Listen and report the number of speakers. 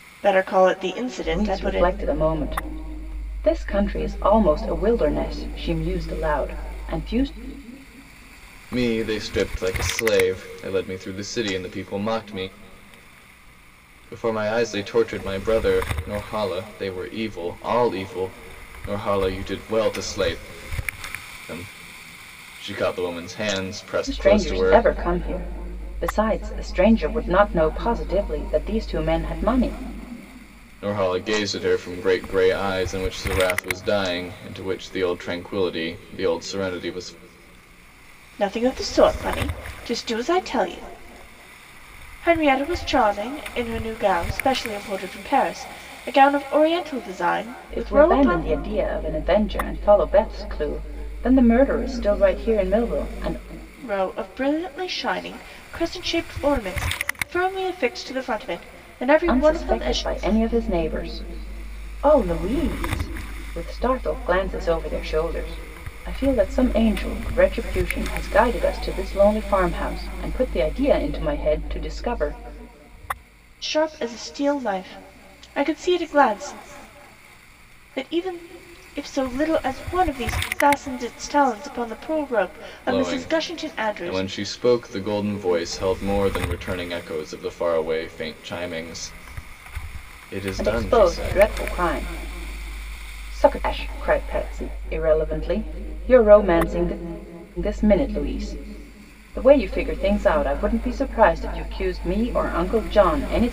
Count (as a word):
three